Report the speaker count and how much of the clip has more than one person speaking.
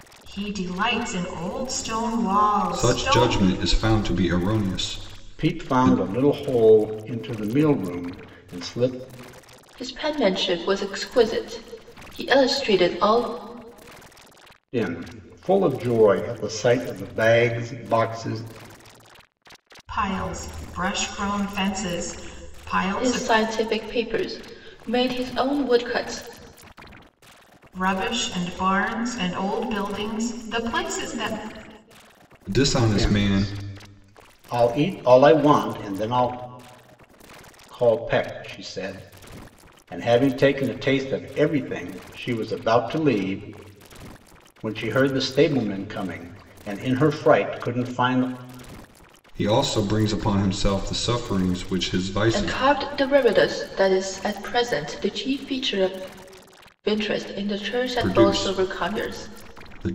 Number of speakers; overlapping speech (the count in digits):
4, about 7%